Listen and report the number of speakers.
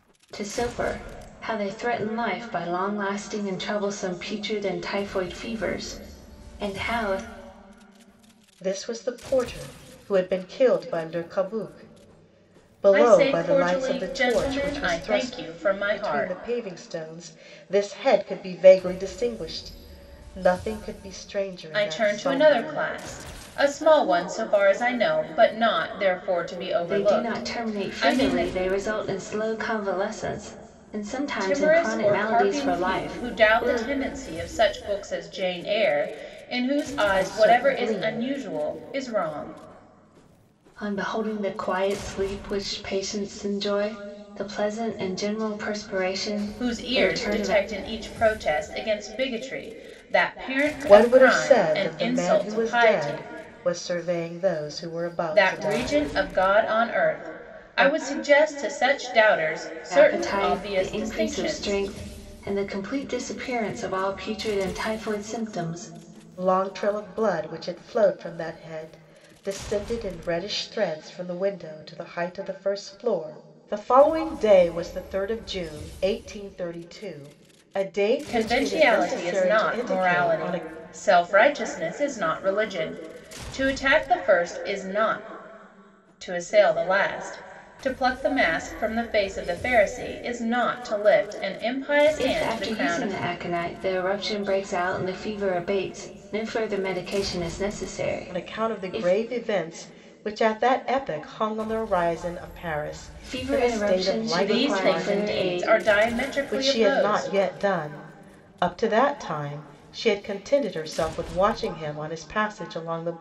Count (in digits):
3